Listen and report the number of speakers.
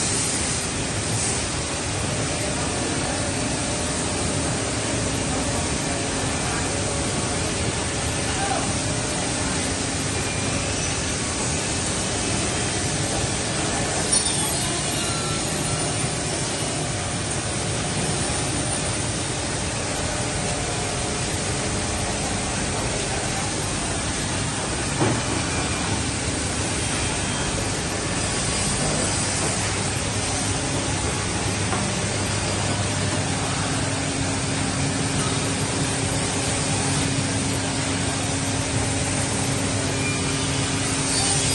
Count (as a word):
zero